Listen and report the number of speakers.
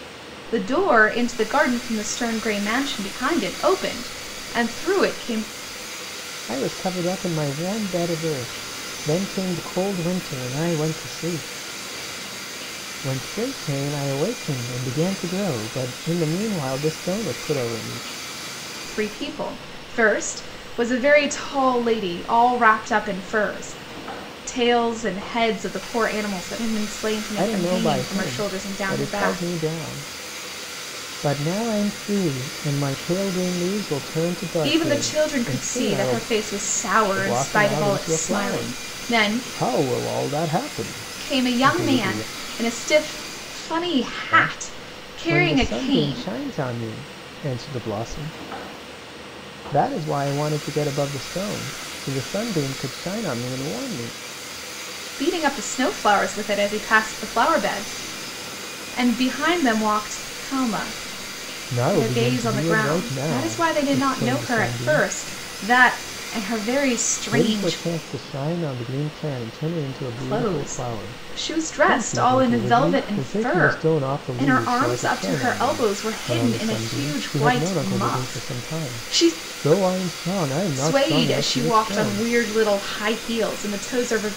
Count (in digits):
2